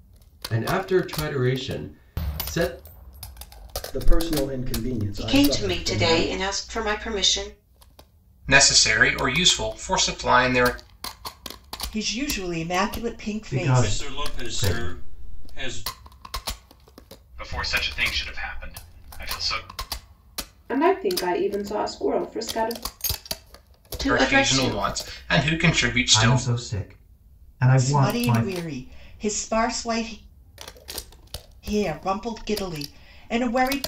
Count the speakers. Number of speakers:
nine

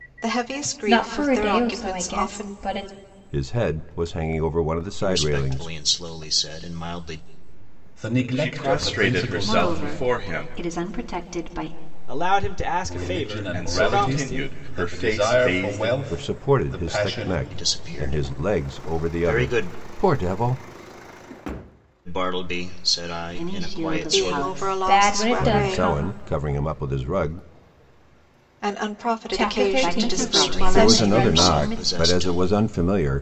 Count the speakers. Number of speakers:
eight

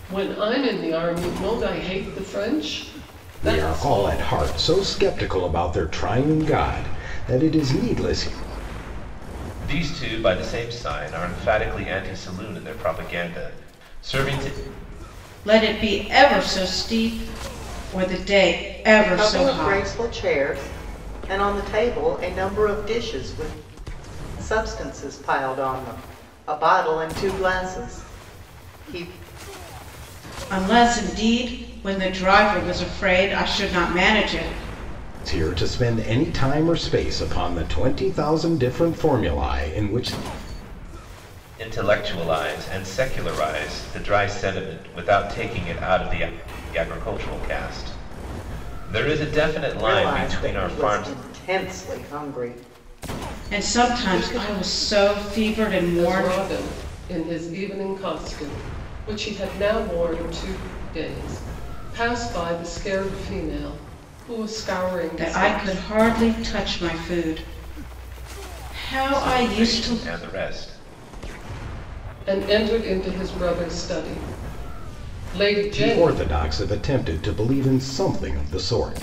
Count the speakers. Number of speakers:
five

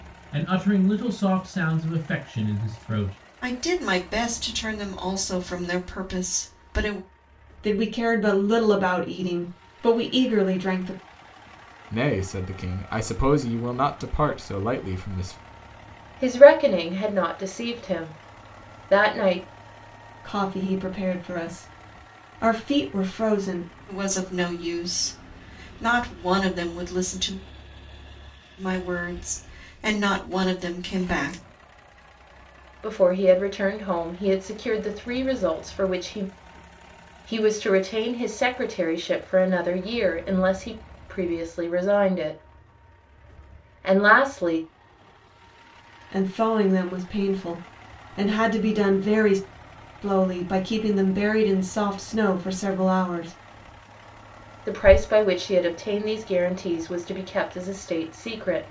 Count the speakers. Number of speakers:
five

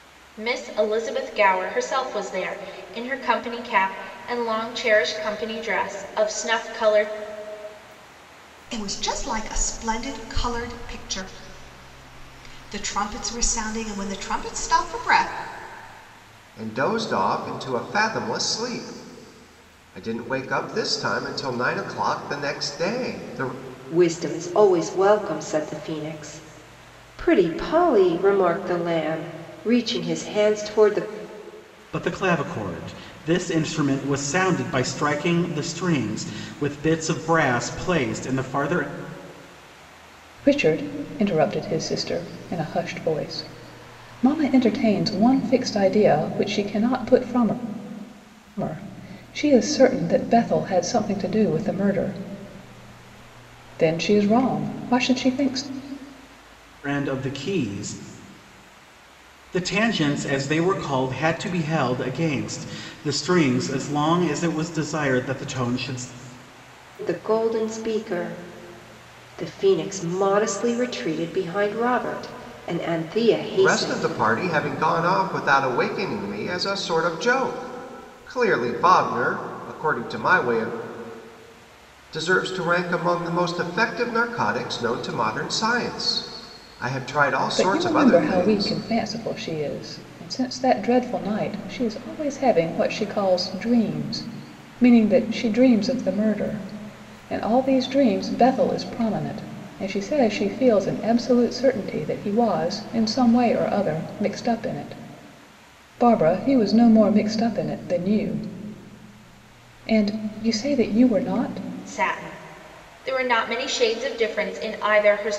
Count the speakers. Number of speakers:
six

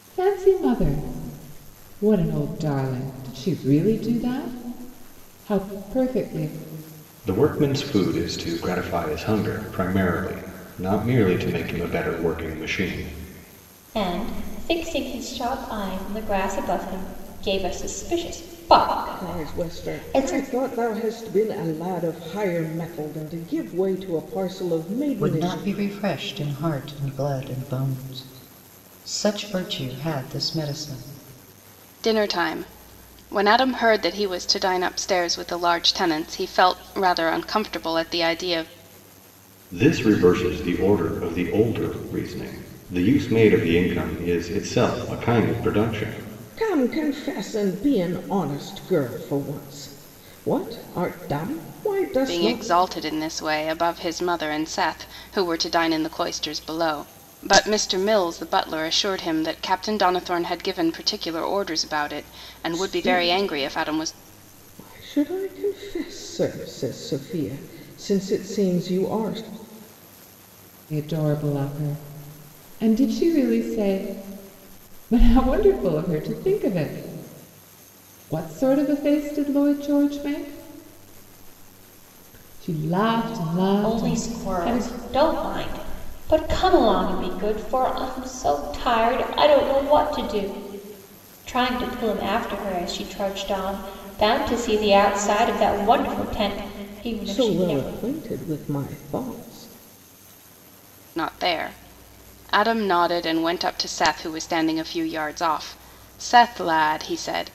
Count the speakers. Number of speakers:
six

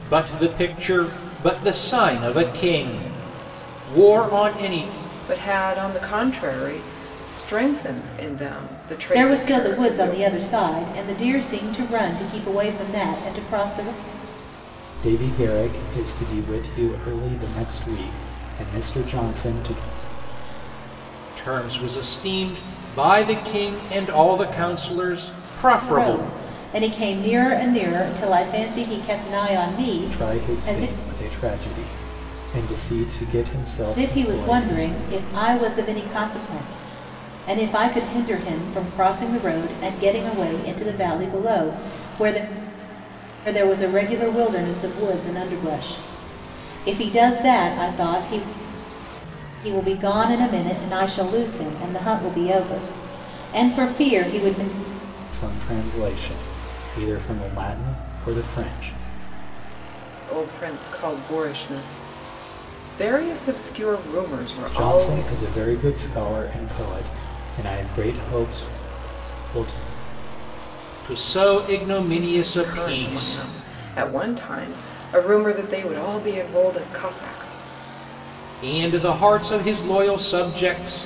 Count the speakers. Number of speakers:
four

